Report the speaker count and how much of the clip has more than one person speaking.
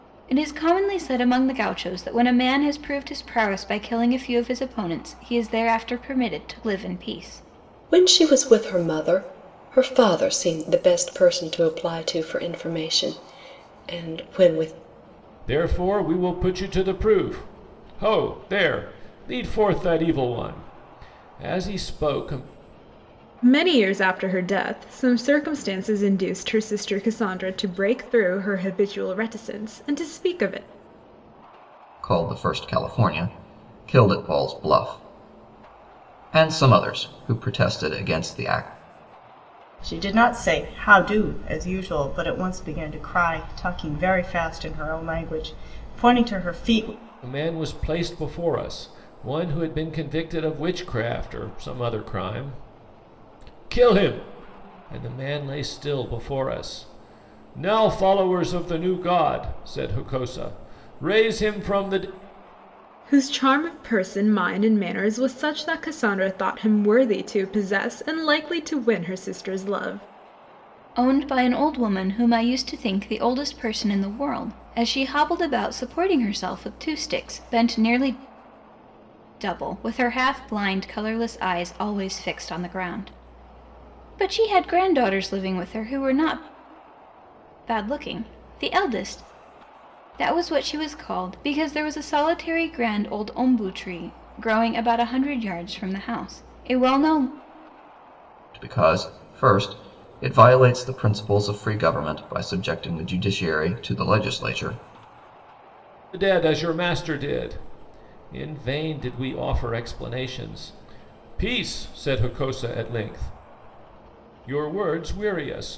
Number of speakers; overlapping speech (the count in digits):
6, no overlap